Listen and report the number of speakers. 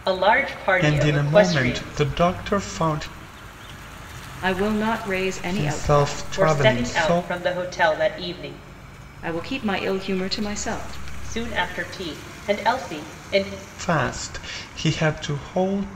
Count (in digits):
3